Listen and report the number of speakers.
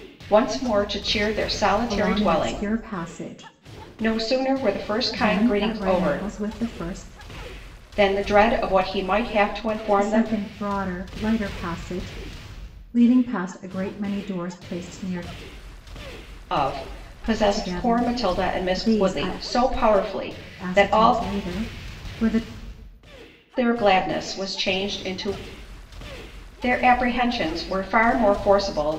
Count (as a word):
two